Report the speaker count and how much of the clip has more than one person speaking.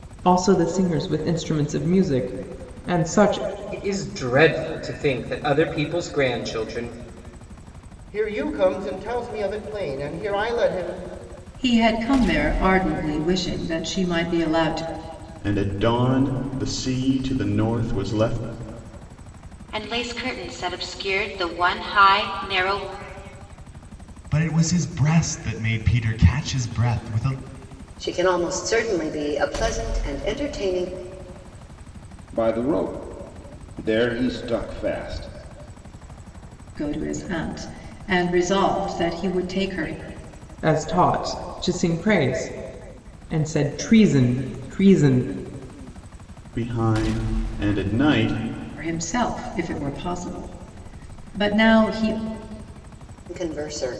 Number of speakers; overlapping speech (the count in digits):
9, no overlap